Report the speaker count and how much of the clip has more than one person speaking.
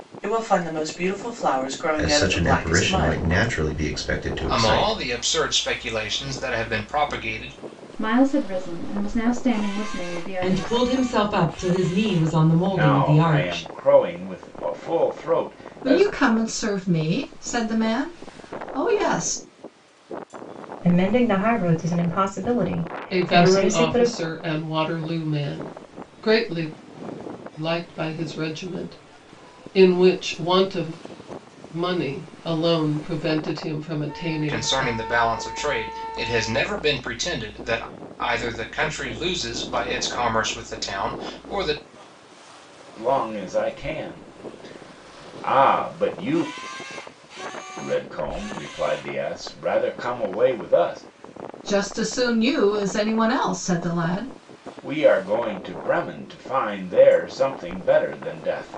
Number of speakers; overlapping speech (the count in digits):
9, about 9%